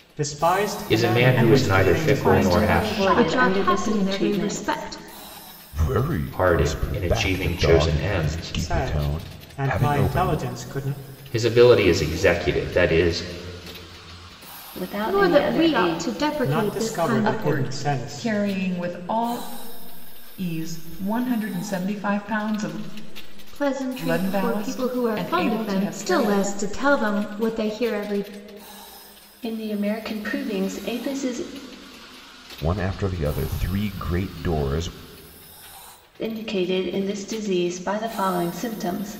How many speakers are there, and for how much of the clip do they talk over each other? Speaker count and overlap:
6, about 34%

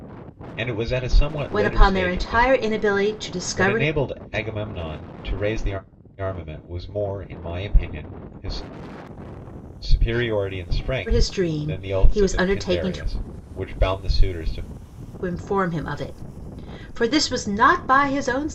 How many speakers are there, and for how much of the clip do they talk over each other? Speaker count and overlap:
2, about 19%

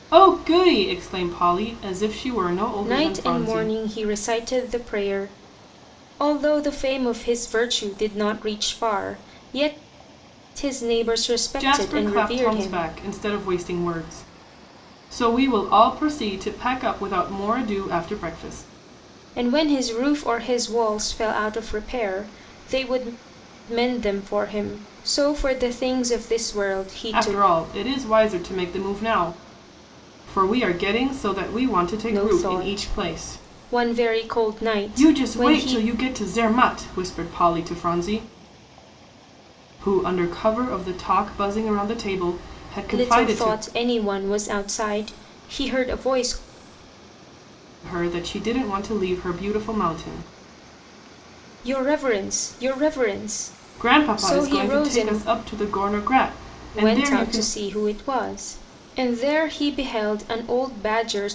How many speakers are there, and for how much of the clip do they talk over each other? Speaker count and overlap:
2, about 13%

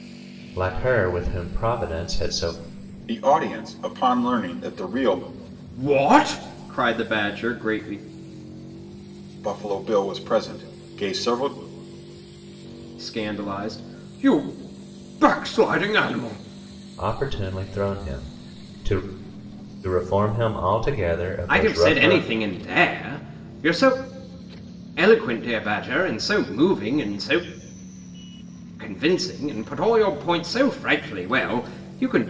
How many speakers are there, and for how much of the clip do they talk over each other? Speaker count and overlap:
3, about 2%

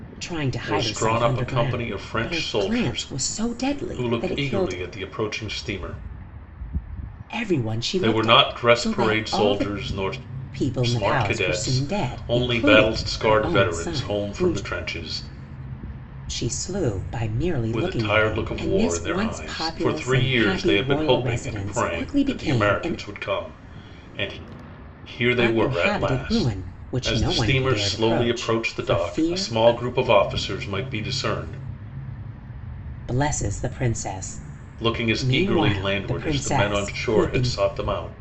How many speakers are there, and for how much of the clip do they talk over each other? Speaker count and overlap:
2, about 55%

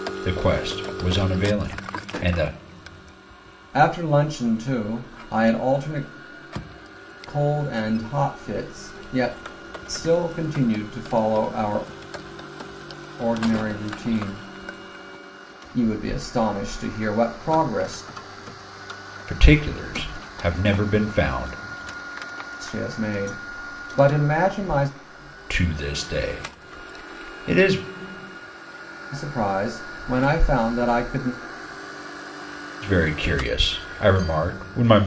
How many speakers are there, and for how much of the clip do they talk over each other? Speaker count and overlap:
2, no overlap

